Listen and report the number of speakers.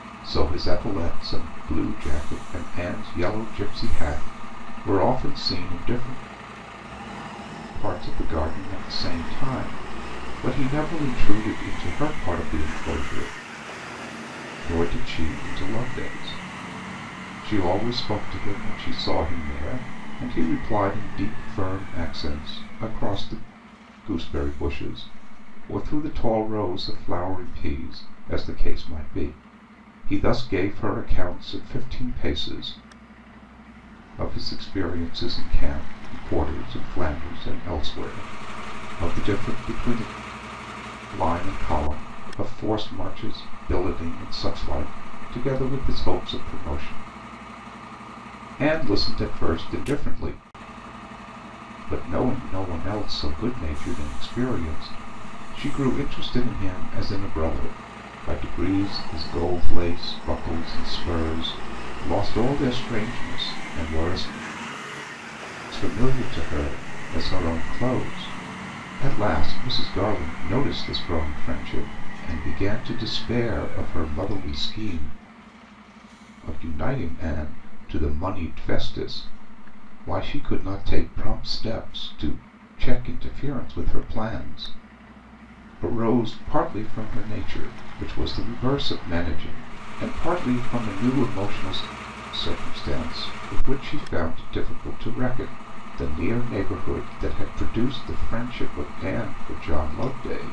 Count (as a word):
one